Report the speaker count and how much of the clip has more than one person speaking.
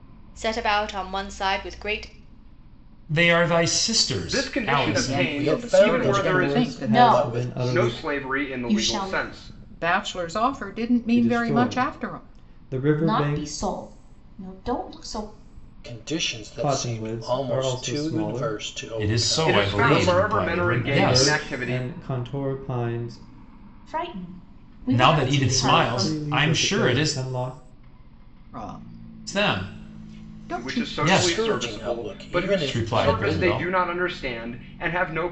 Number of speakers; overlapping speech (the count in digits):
7, about 51%